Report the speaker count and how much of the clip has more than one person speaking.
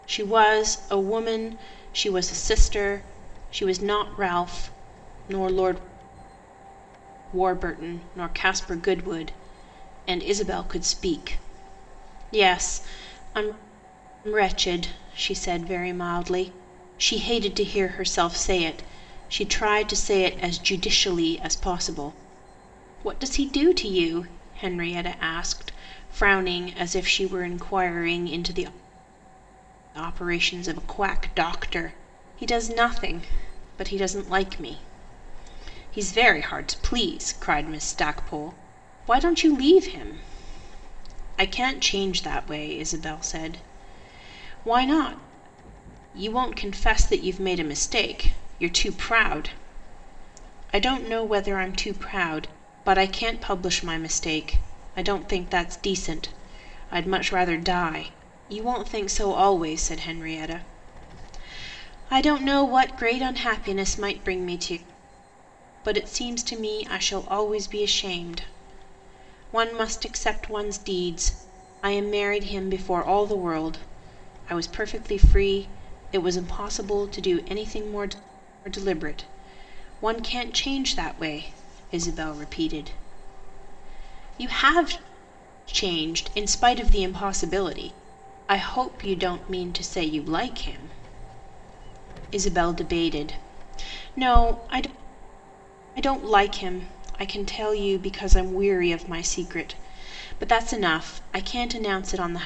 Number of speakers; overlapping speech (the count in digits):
1, no overlap